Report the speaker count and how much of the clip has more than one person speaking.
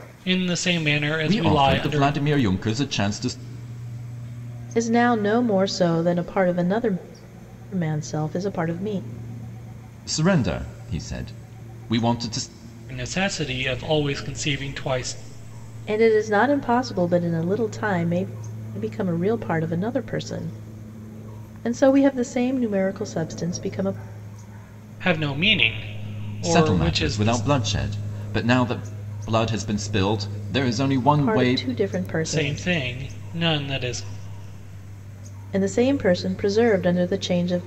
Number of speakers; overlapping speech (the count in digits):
3, about 8%